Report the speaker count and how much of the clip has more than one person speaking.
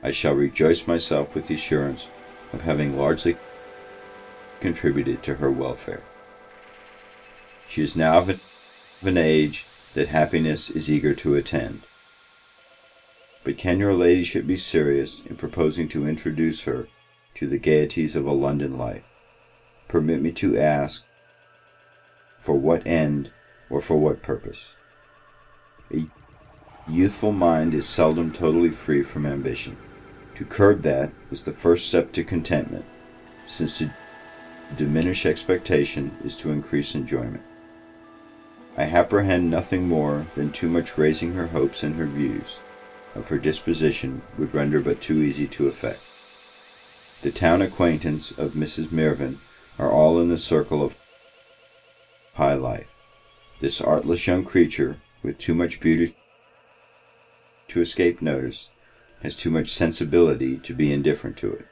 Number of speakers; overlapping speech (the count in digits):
1, no overlap